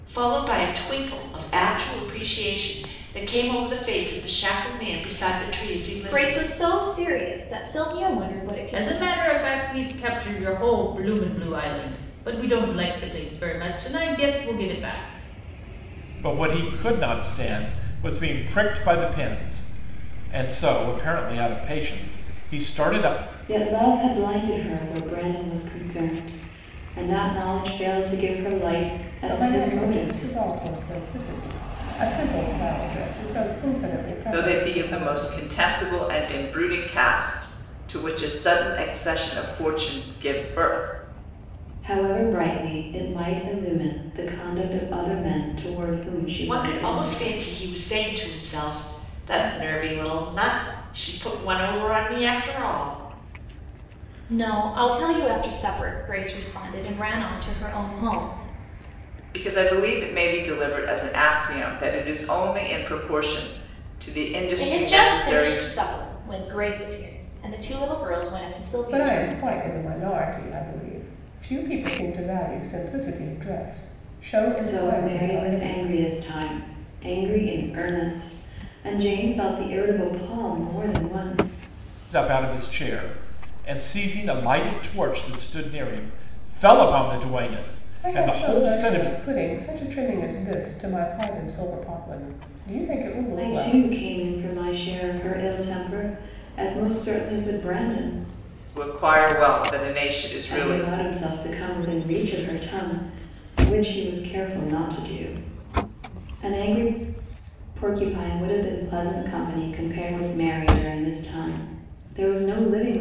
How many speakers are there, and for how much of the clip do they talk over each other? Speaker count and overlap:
7, about 8%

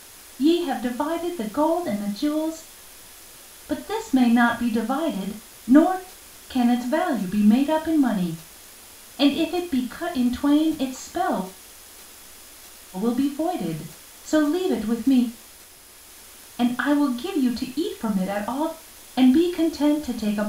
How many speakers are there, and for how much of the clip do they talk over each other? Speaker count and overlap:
1, no overlap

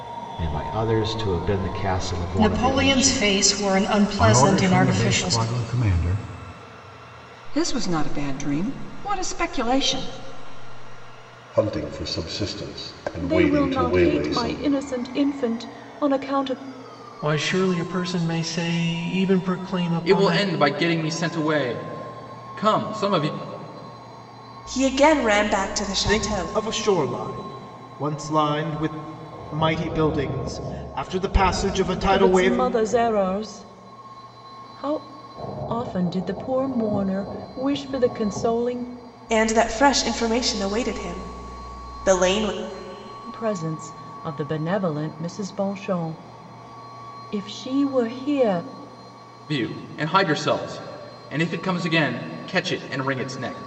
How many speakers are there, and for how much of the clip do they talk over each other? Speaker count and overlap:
10, about 10%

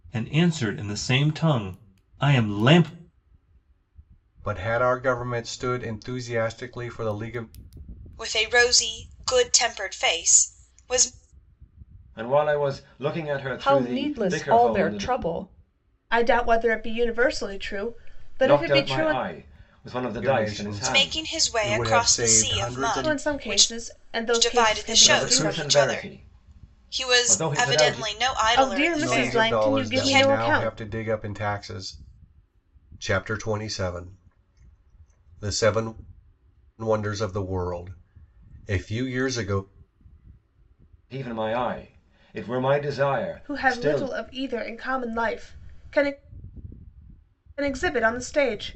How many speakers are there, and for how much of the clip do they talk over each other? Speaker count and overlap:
6, about 26%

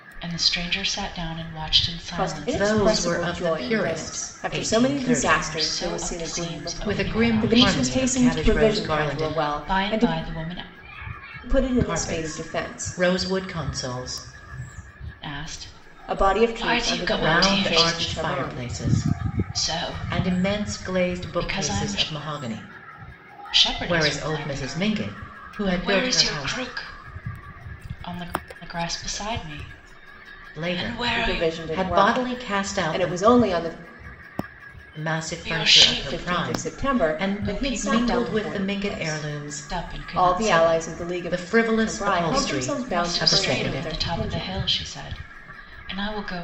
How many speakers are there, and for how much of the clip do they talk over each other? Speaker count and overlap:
3, about 60%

